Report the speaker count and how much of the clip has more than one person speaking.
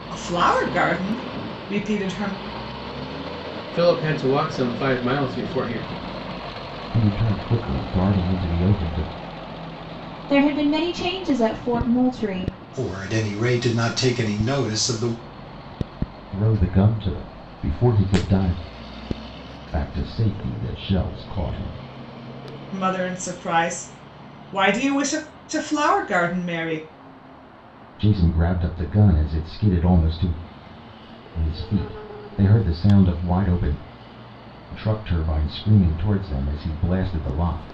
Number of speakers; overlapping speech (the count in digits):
5, no overlap